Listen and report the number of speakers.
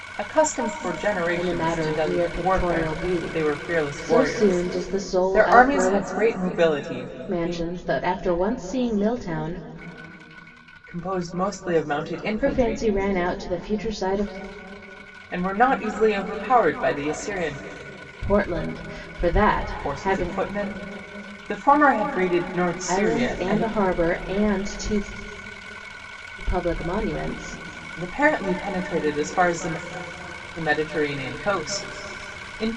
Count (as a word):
two